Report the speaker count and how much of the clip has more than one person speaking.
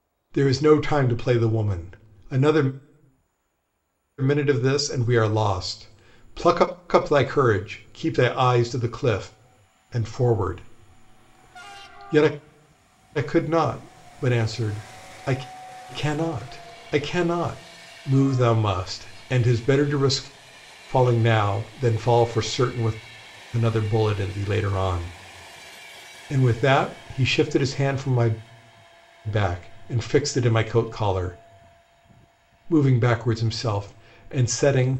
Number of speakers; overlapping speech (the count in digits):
1, no overlap